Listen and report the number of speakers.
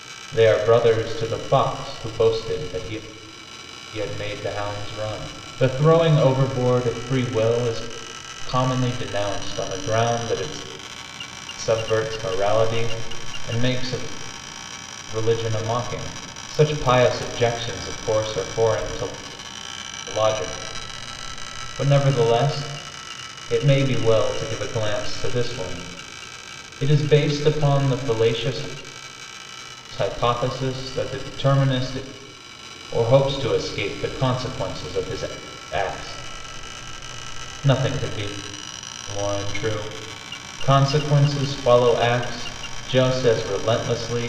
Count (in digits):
1